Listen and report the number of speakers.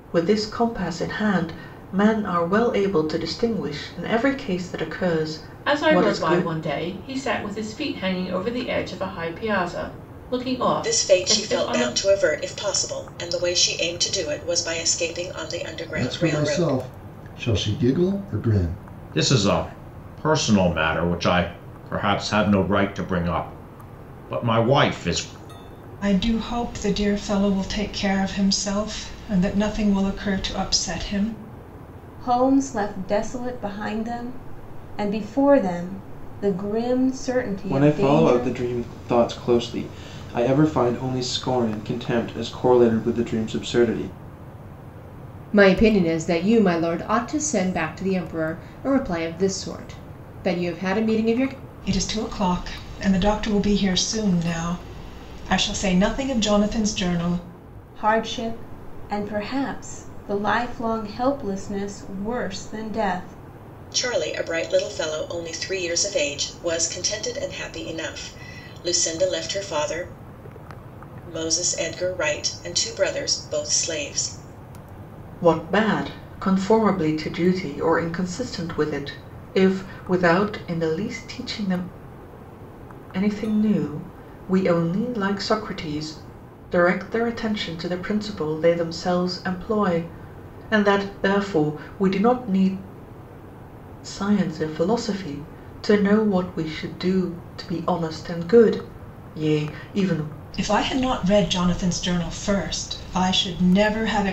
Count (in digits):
9